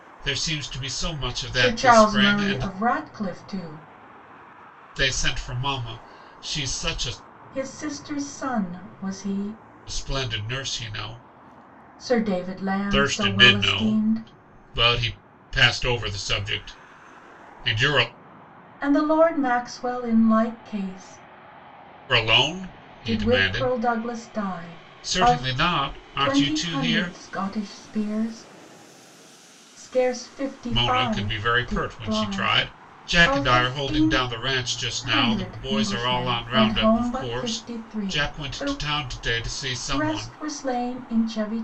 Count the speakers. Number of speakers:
2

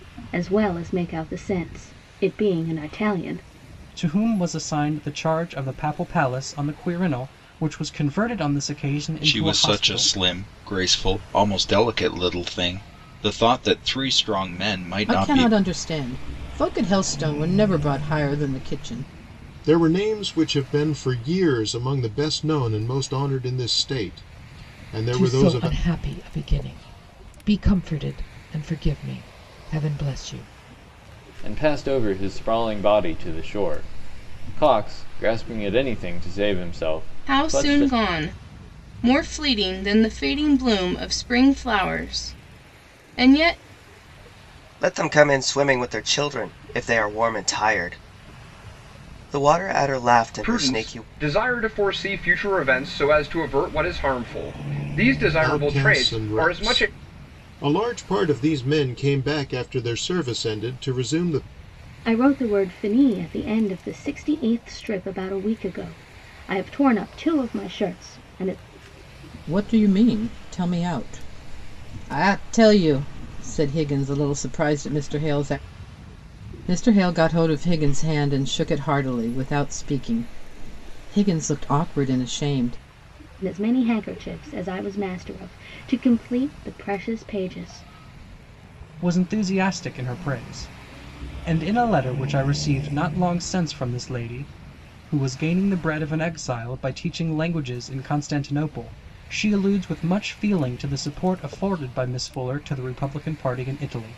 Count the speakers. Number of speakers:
10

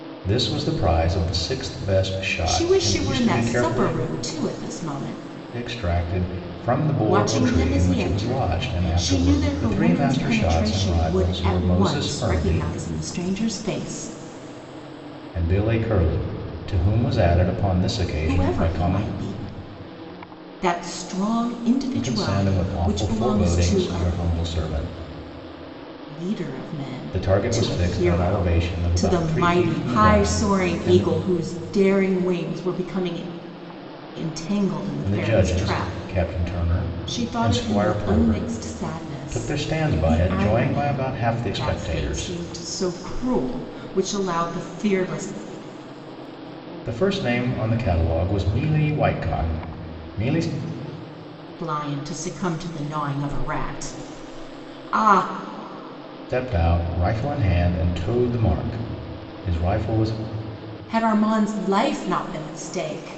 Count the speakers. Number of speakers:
2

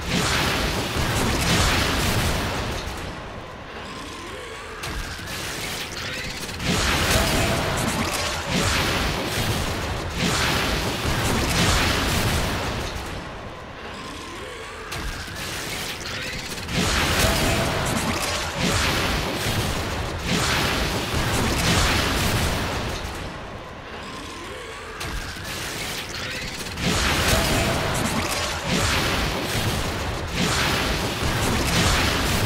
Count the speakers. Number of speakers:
0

